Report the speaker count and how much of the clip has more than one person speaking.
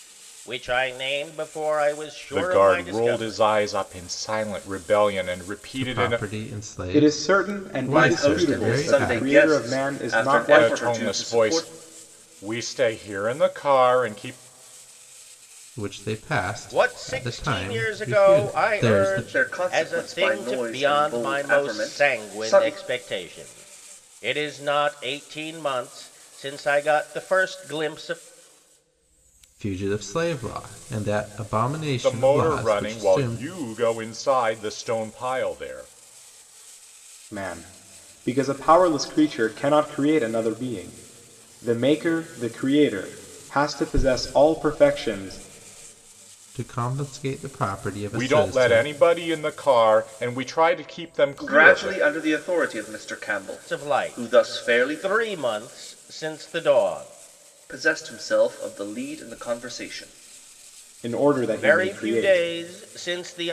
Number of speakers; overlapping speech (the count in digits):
5, about 28%